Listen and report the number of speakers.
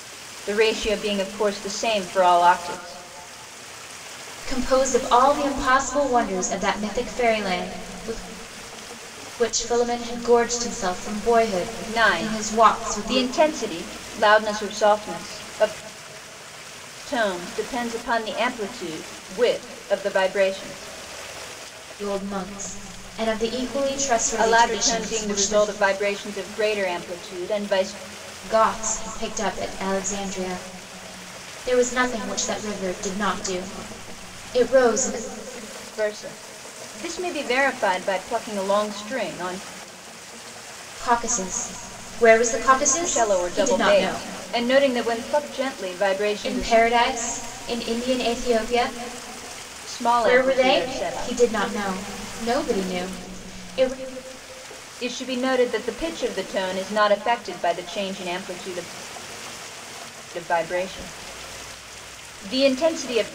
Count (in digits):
2